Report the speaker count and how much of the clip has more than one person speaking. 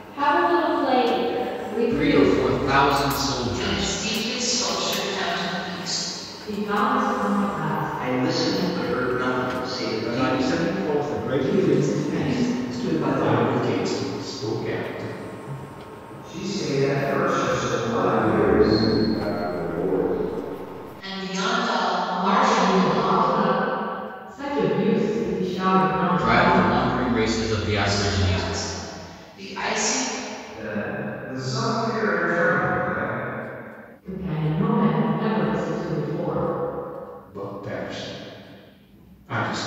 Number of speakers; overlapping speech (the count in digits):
10, about 21%